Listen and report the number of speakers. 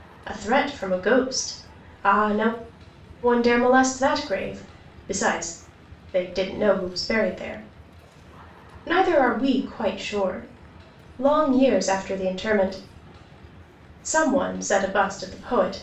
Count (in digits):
1